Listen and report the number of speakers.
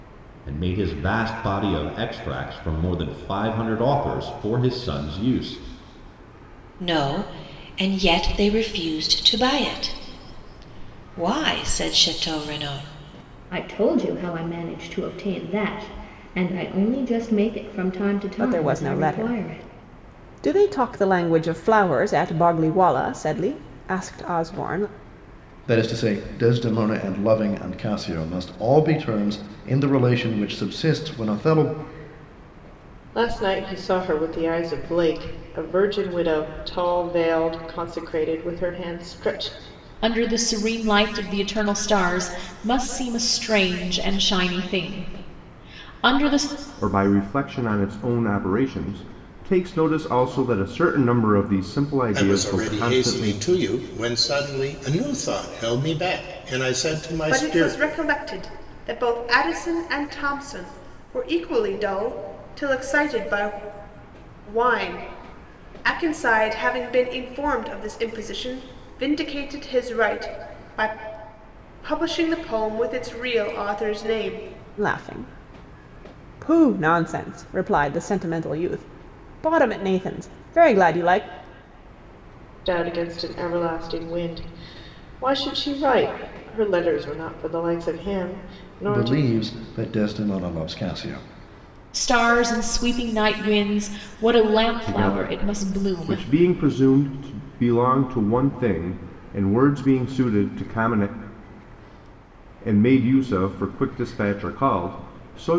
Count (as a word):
ten